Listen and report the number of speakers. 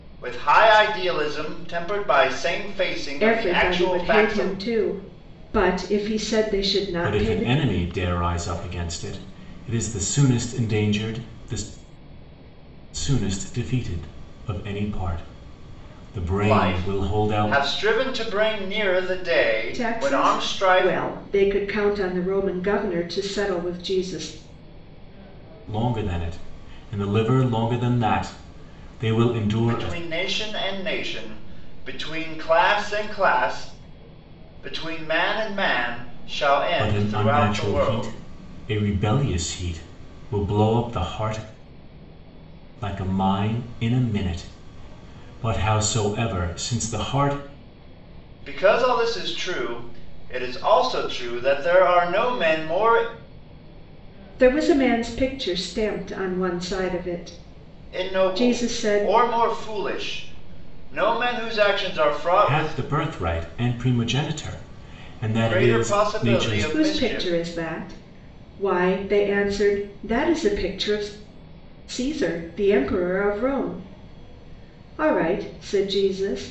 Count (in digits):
3